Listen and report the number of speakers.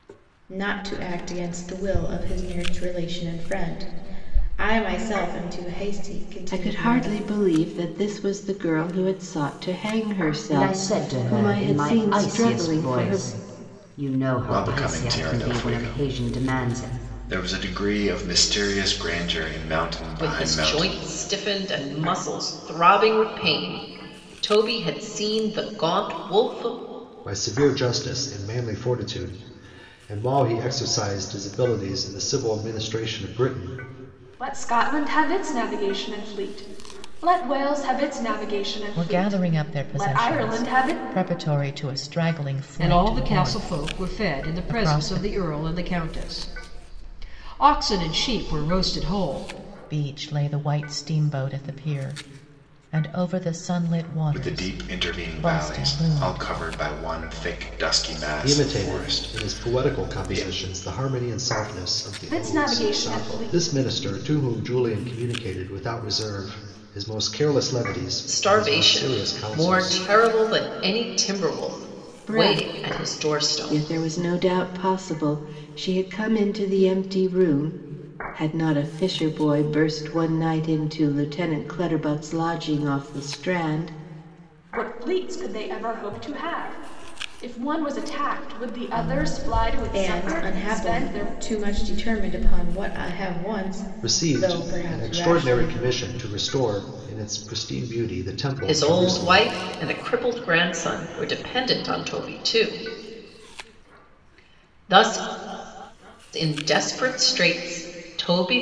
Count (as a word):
nine